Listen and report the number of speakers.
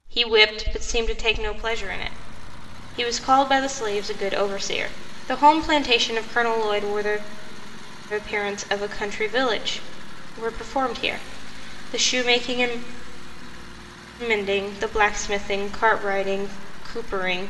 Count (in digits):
1